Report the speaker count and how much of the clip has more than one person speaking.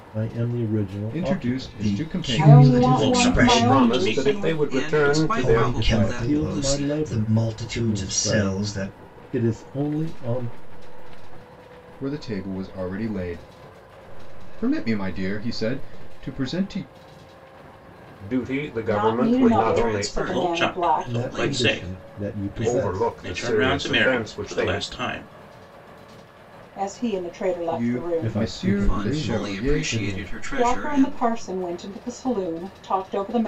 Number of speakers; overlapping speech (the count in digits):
8, about 59%